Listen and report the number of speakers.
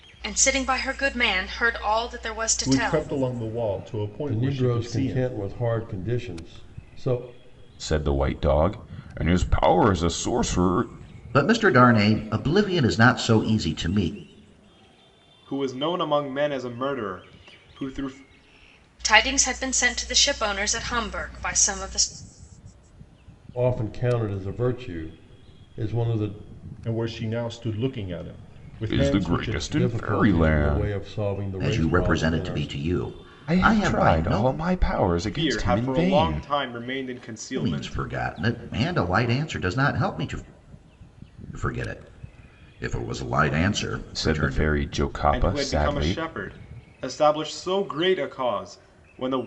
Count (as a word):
six